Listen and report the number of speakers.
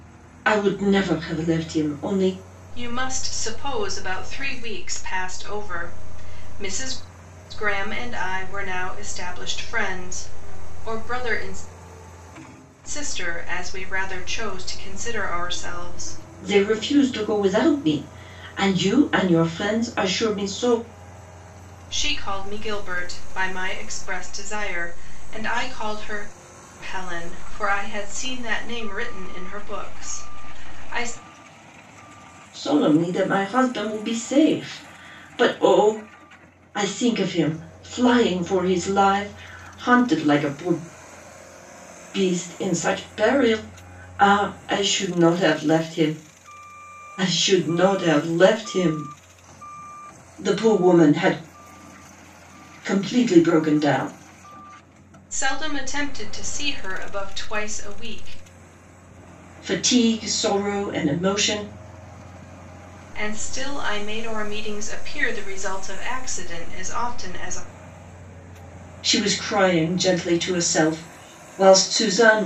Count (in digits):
2